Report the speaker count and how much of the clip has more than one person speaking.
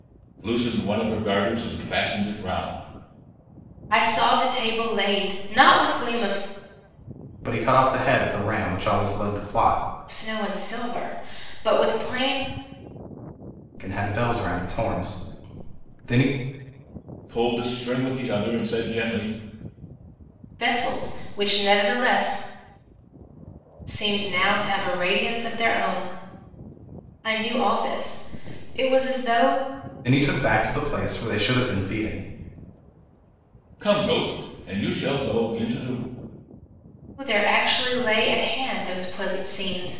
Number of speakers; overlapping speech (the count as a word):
three, no overlap